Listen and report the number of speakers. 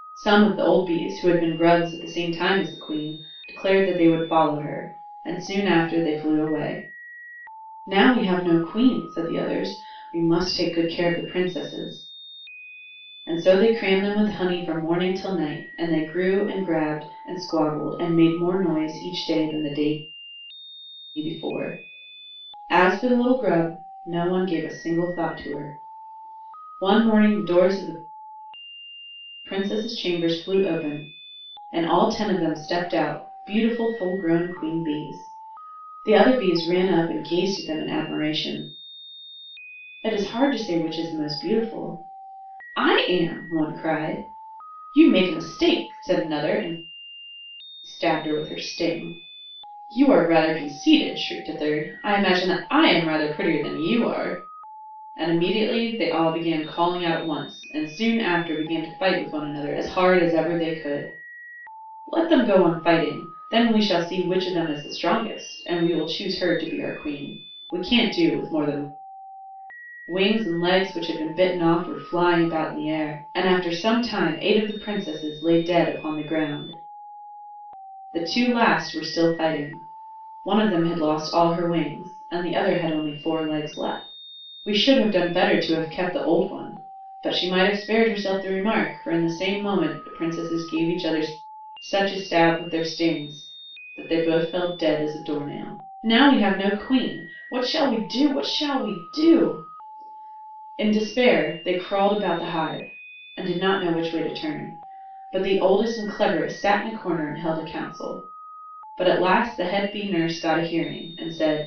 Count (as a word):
one